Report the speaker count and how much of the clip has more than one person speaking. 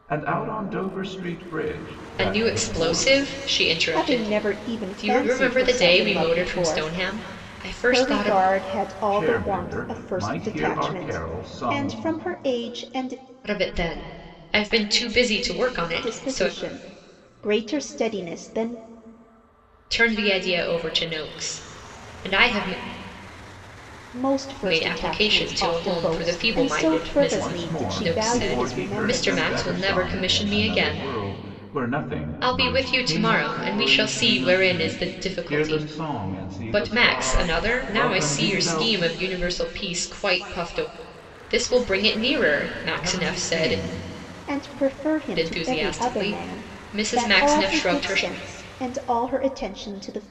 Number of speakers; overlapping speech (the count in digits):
3, about 49%